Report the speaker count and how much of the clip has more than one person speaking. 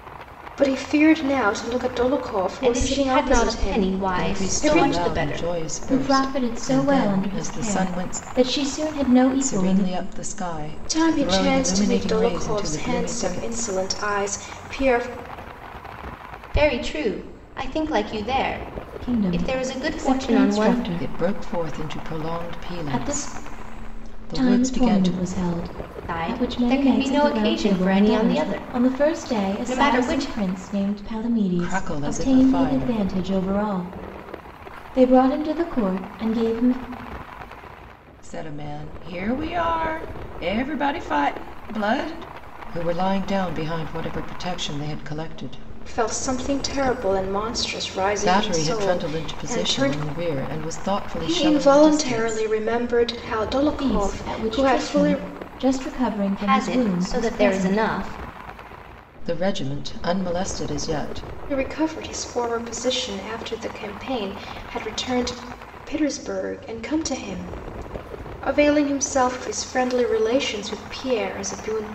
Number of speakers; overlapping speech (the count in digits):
4, about 38%